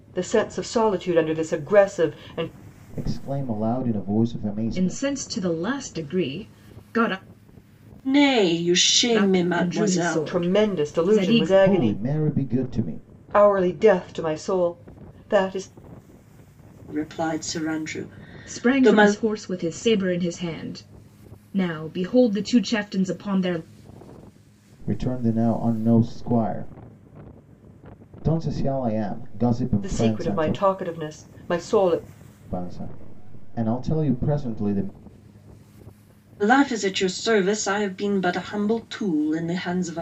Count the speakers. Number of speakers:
four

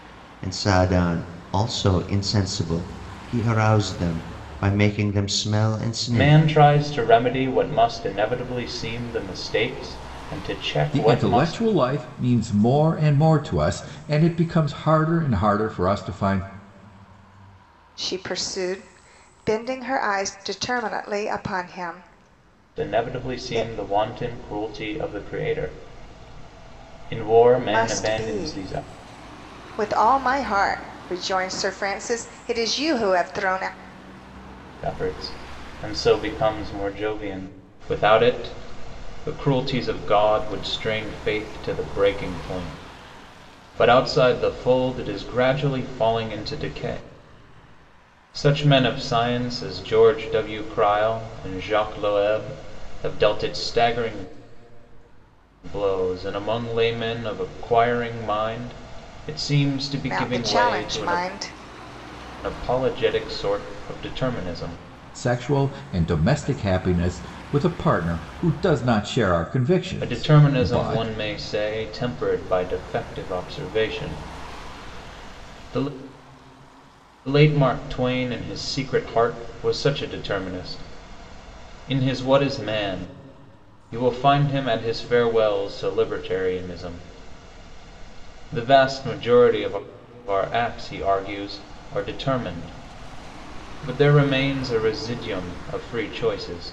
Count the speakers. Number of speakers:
four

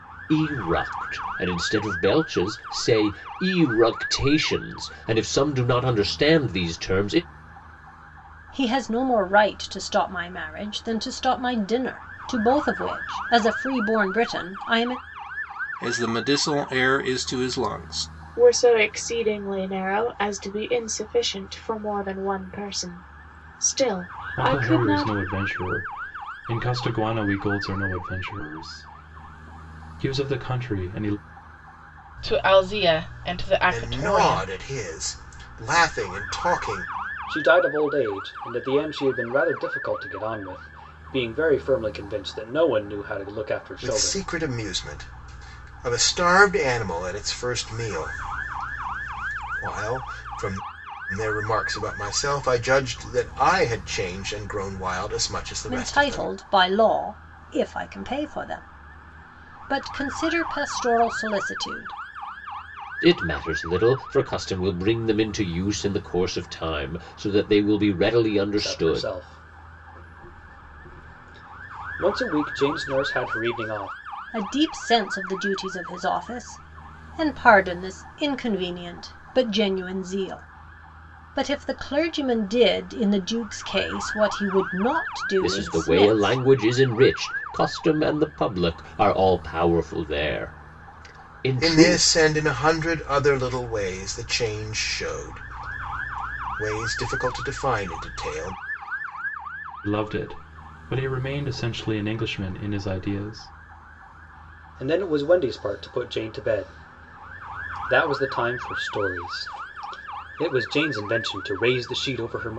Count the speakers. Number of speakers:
eight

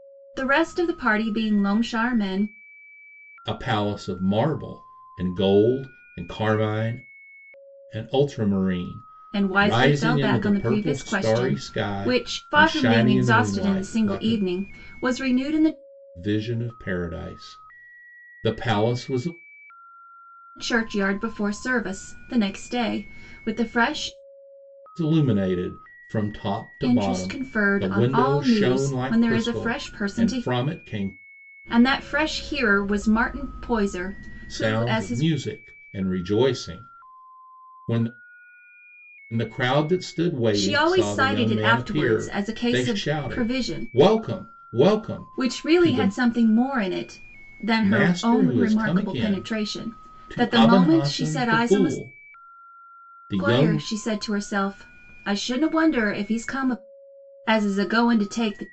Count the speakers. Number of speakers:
two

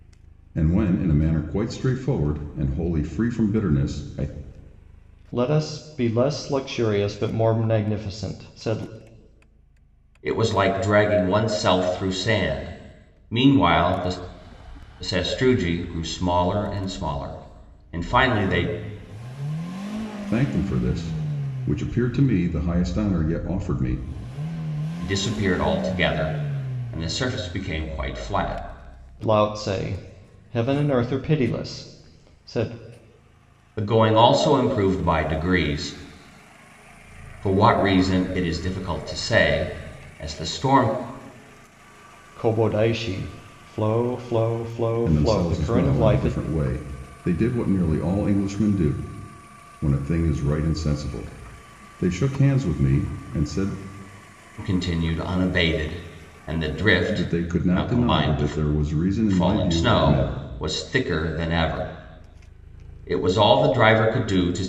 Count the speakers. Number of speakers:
three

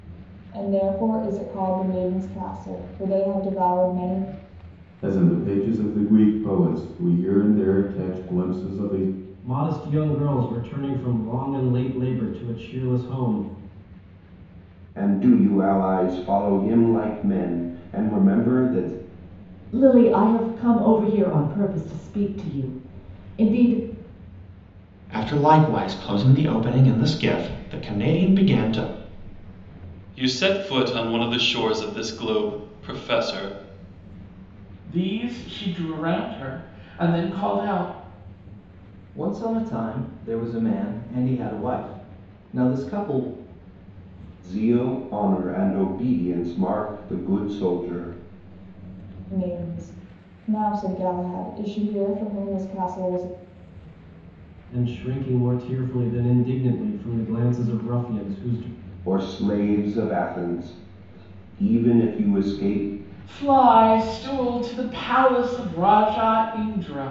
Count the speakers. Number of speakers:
nine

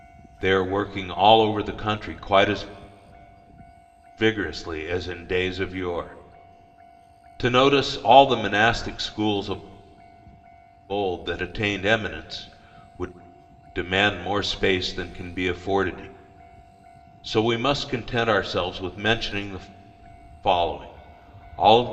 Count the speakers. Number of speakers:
one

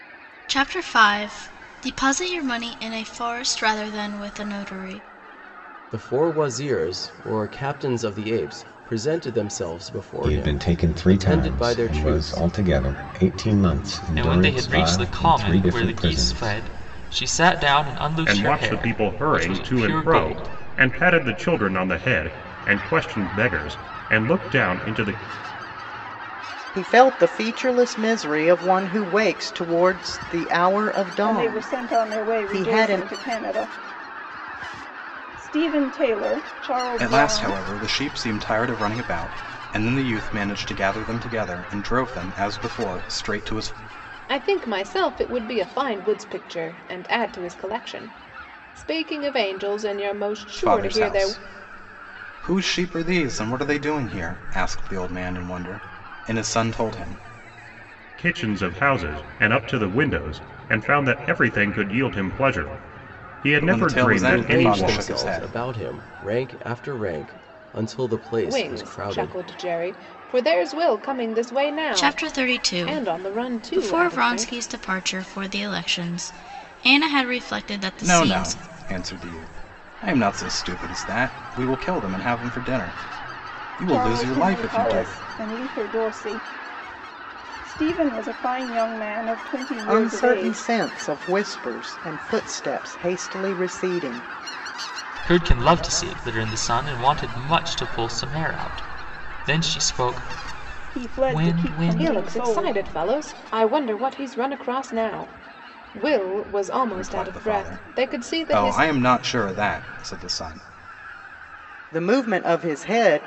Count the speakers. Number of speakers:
nine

